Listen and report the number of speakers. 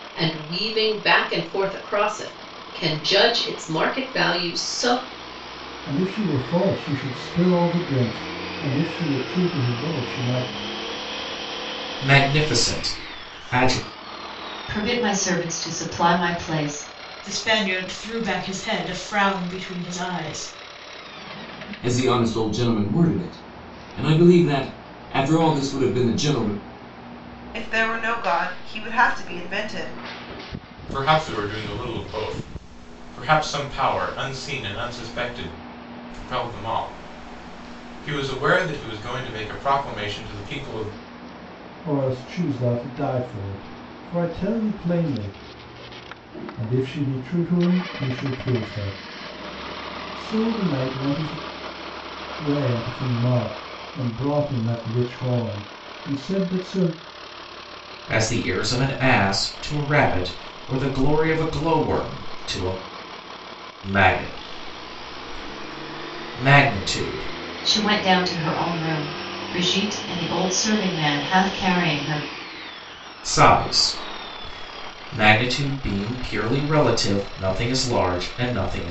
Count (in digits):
8